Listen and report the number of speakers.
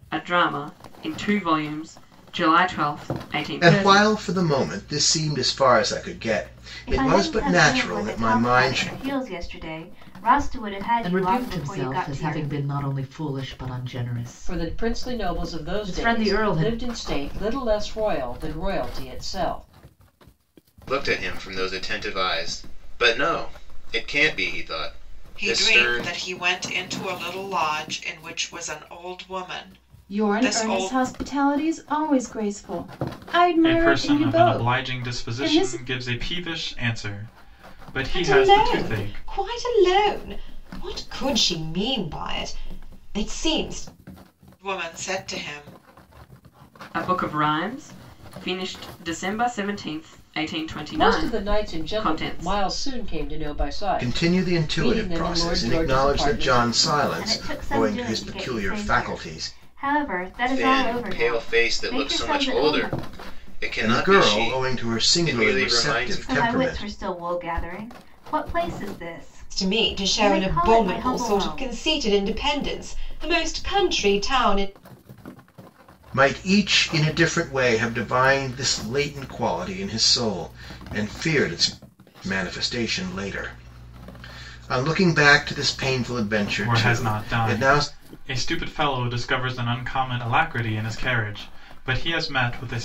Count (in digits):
10